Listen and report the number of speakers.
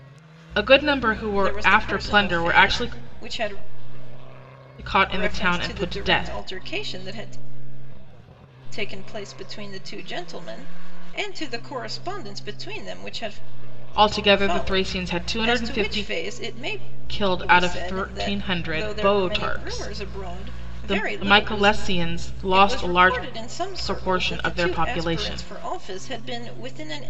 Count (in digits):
2